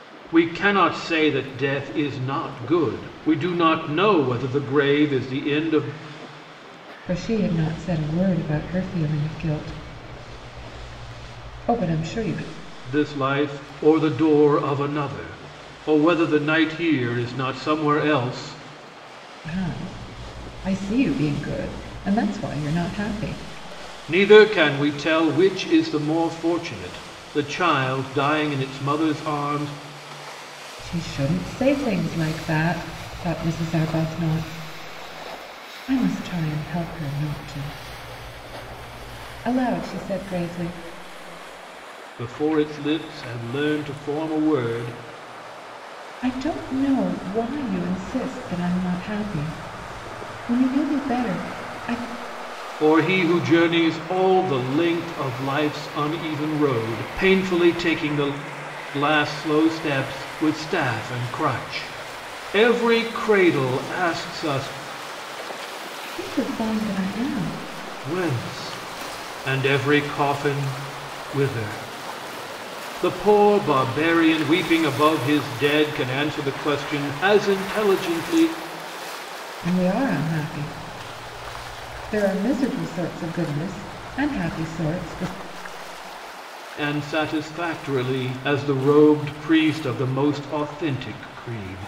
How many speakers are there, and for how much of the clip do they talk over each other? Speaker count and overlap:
2, no overlap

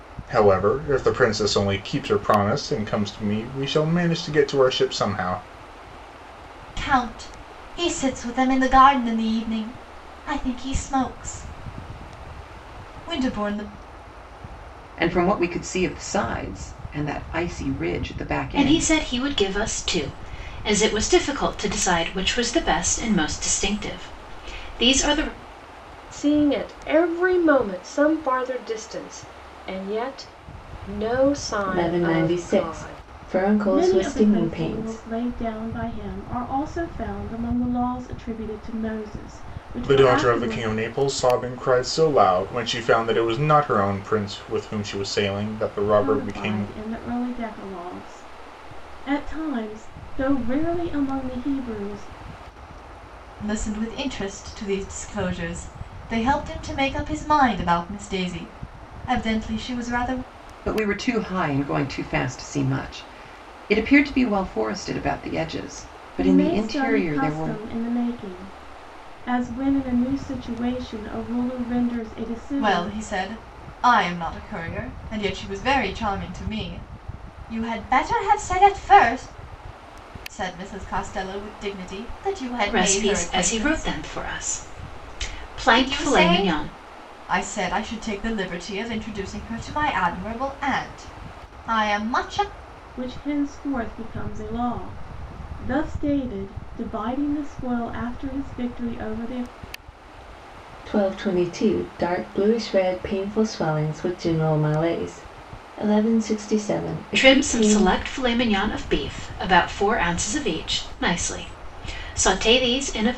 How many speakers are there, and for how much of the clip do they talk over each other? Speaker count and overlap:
7, about 9%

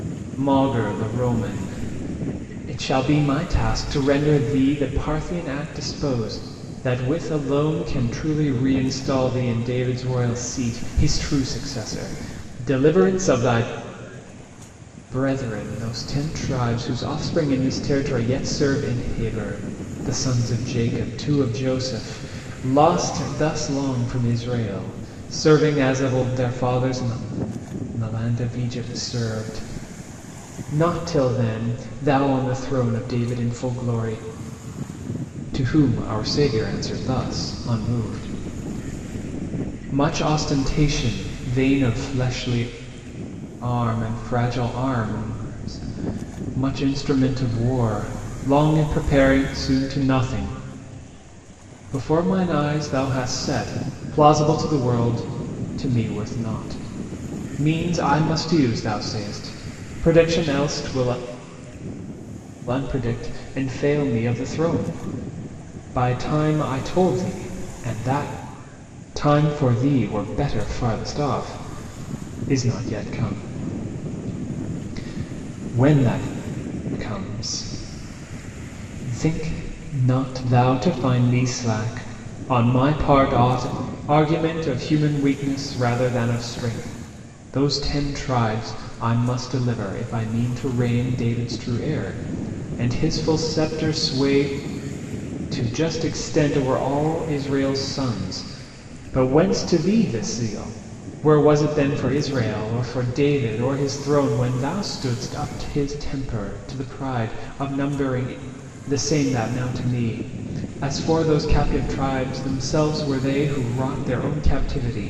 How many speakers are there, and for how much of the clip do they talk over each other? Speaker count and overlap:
1, no overlap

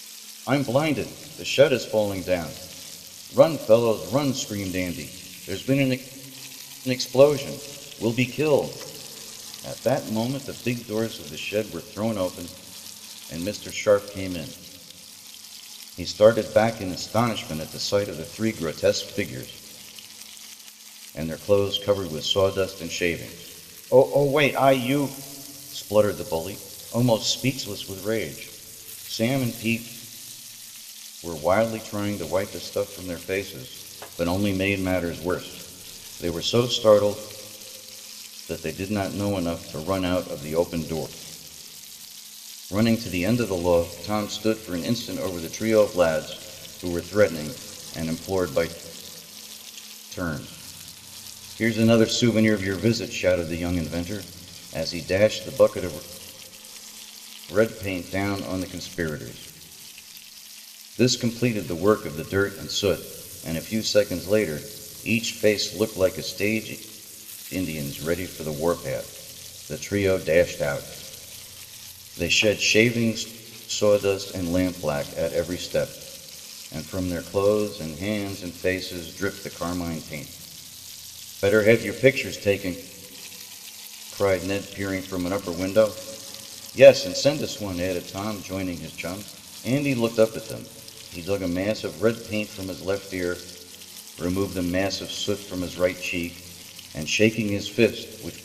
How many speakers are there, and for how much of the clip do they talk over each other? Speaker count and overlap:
1, no overlap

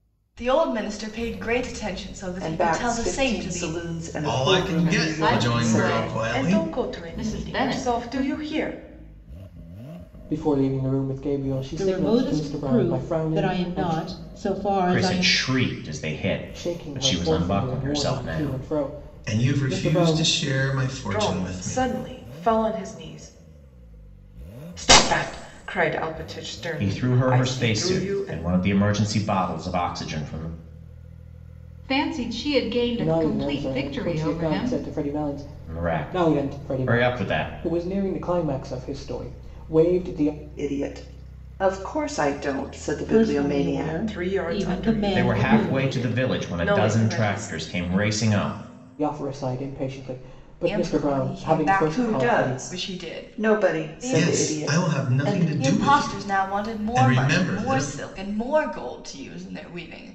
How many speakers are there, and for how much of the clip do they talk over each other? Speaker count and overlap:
8, about 49%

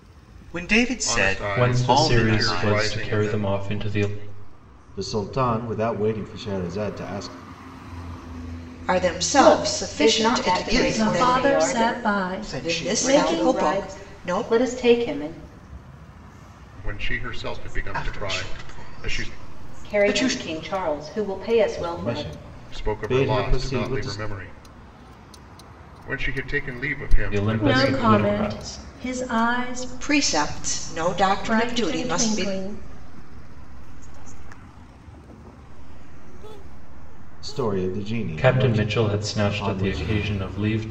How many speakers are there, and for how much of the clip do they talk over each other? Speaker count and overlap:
9, about 51%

